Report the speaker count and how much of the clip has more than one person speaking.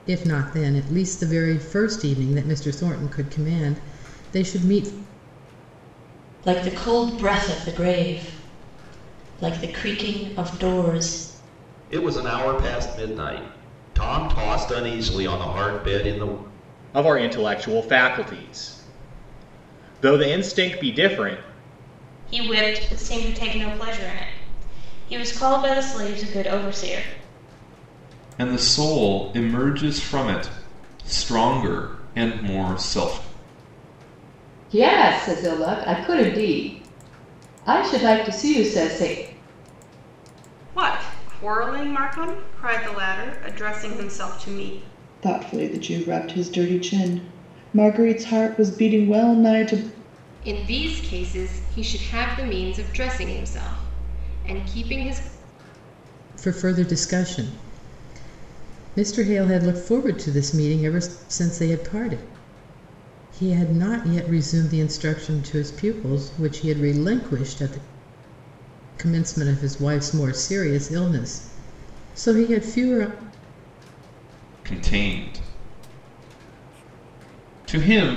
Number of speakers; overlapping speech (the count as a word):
ten, no overlap